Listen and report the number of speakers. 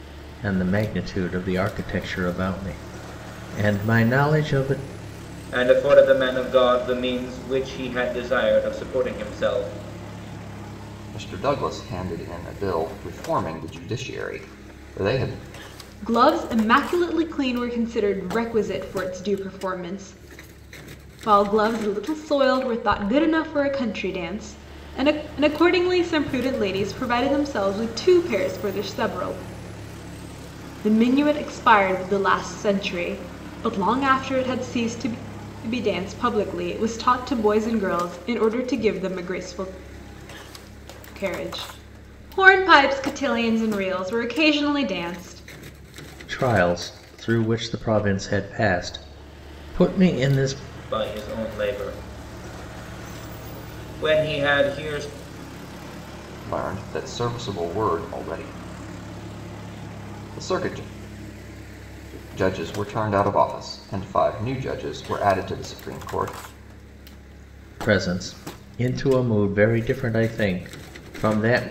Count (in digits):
4